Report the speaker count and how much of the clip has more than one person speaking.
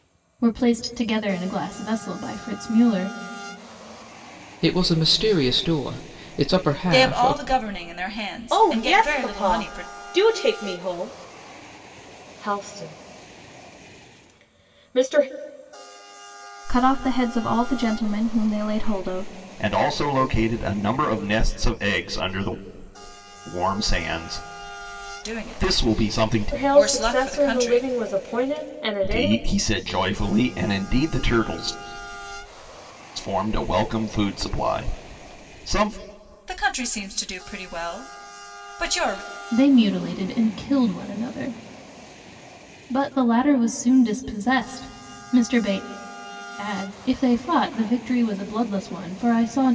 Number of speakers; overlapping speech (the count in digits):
7, about 10%